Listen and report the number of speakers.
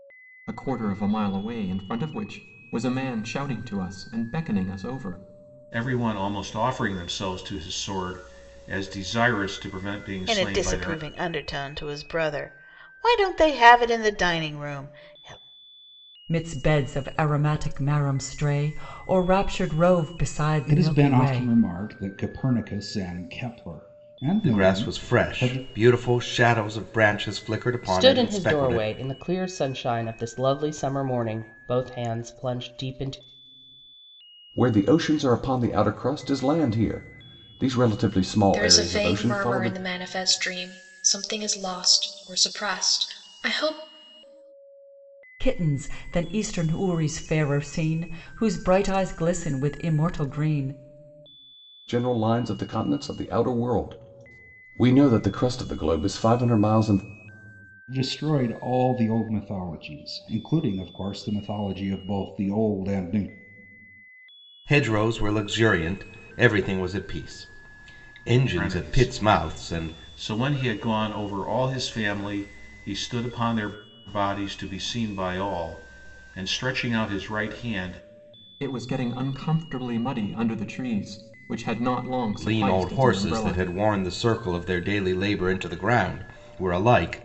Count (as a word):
nine